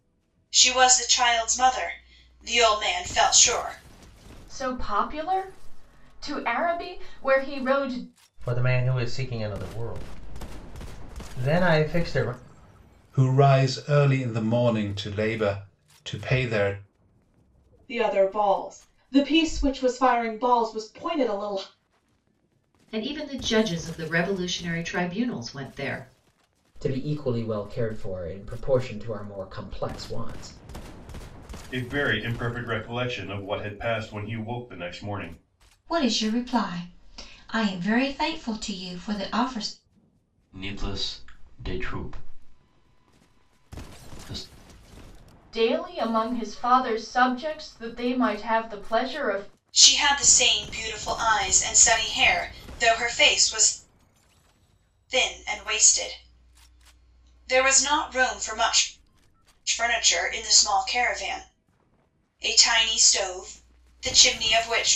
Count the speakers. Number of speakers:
10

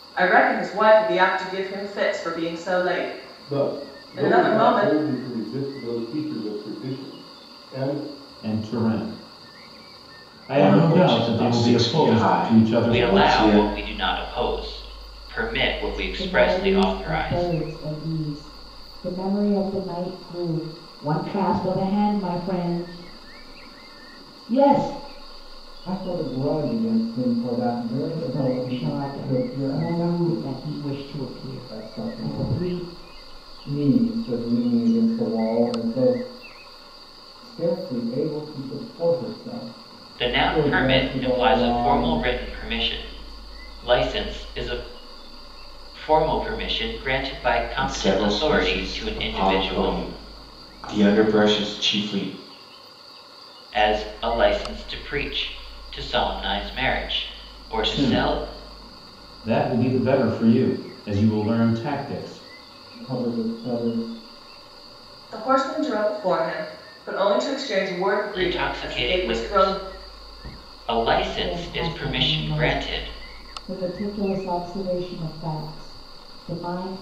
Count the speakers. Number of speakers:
8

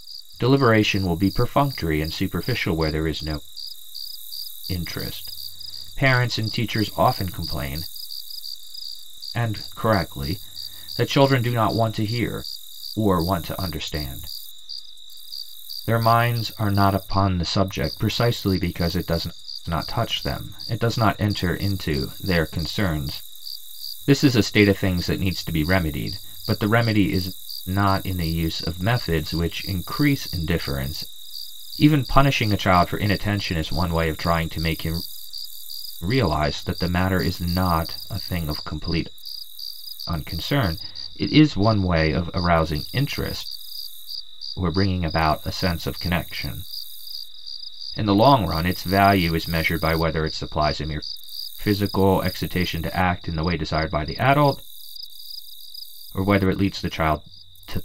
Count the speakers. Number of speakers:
1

